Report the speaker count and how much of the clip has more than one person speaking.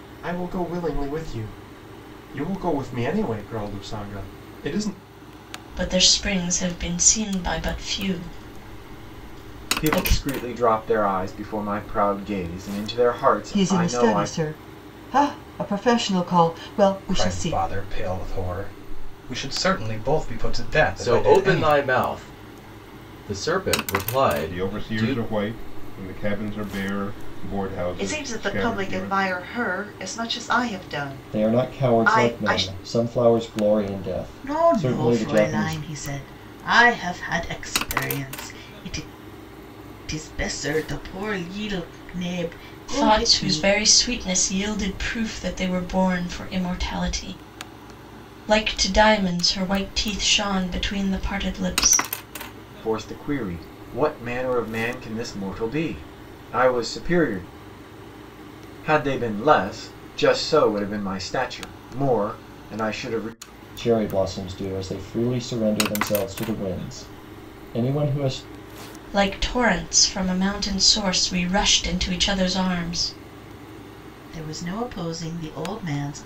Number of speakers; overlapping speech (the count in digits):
10, about 11%